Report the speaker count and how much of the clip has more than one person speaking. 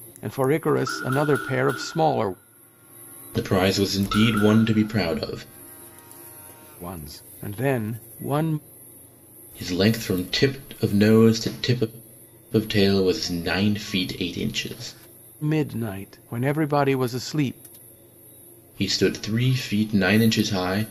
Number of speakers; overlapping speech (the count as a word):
two, no overlap